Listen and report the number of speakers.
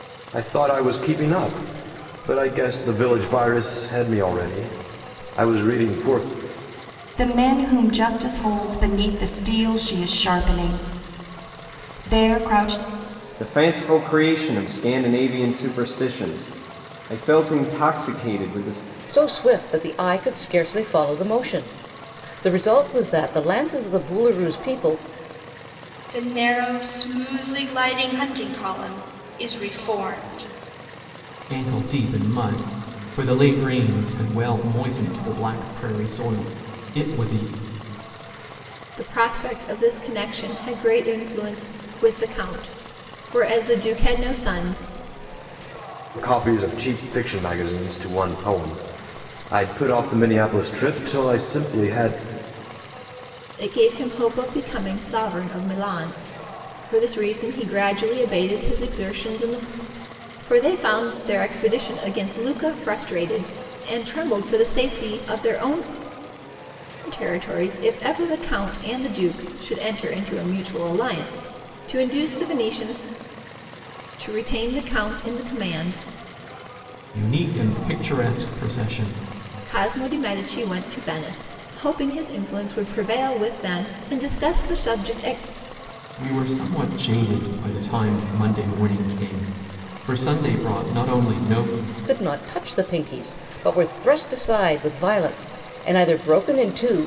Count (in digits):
7